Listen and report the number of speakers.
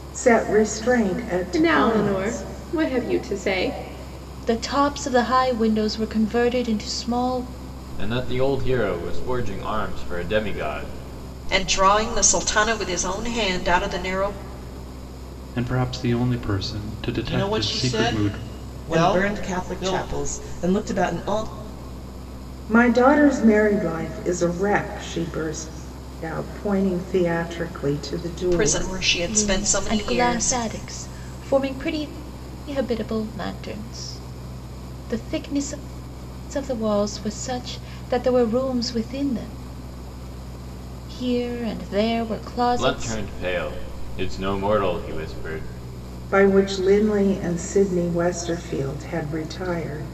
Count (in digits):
8